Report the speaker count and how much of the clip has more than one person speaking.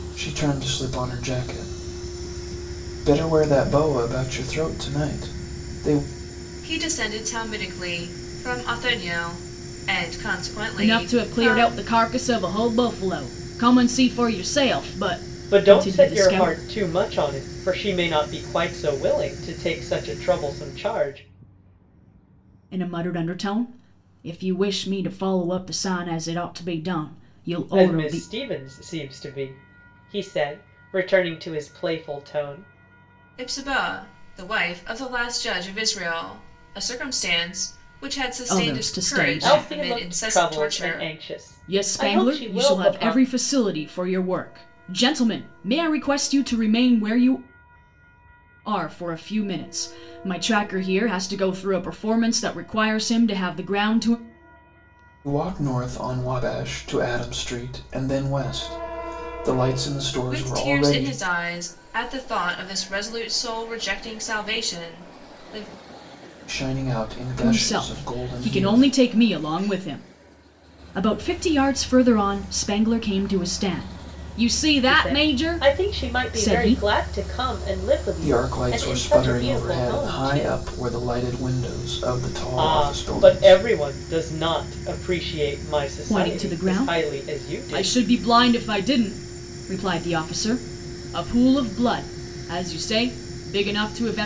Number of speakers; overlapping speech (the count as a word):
four, about 18%